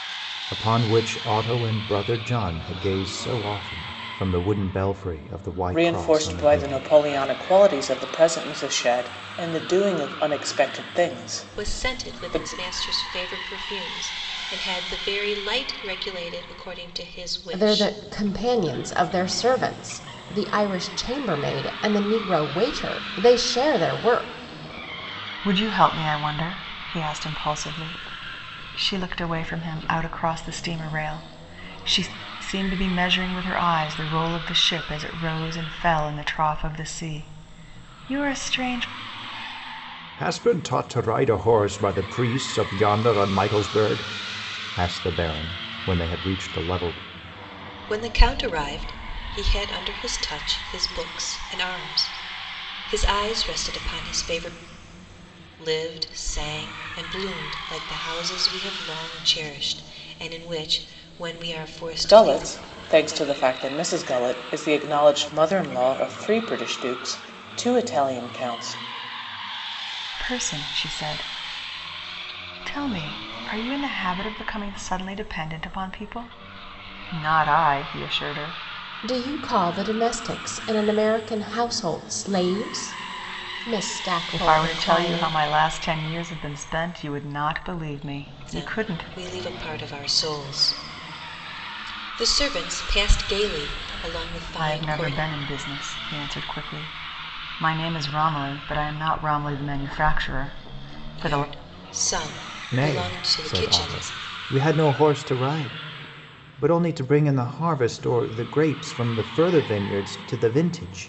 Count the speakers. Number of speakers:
5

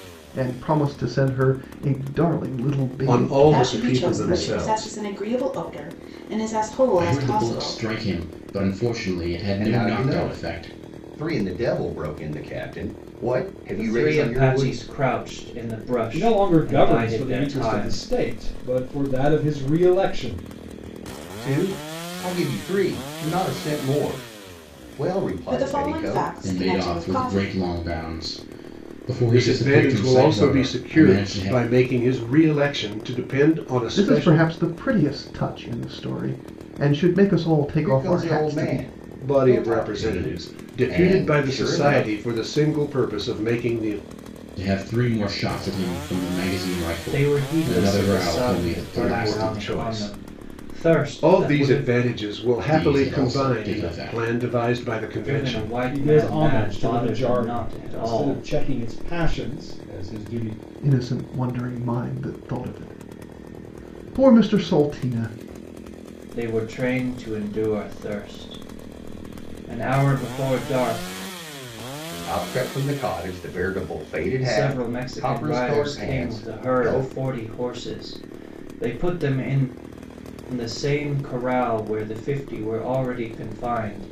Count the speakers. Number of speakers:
7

